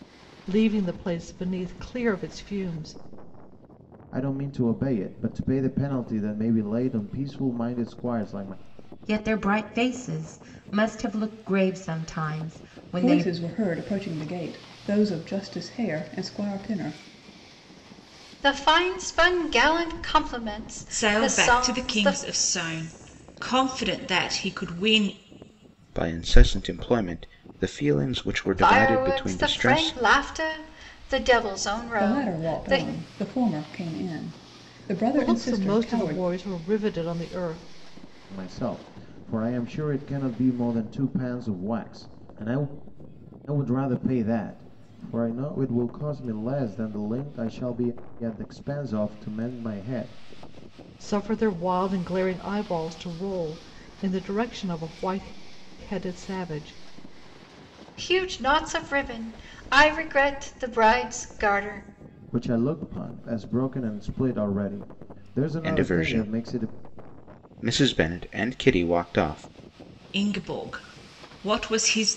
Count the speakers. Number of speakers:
seven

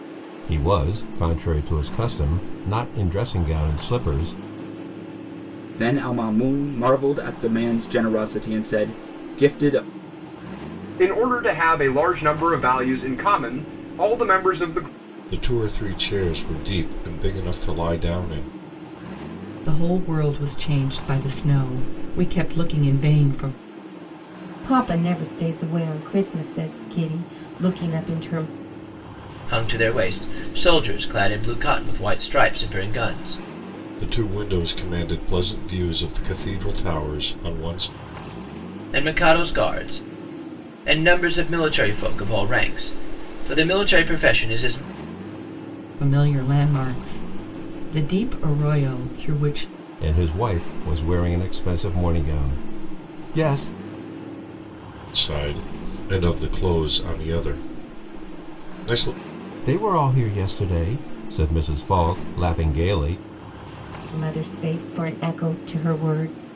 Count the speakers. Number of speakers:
seven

